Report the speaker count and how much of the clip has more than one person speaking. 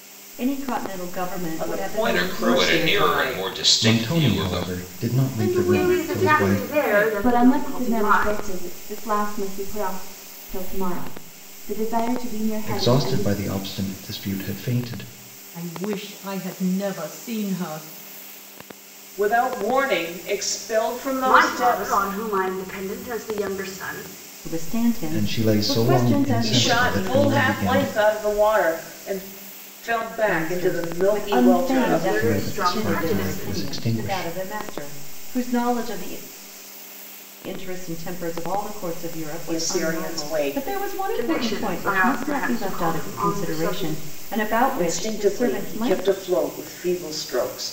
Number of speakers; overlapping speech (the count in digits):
7, about 42%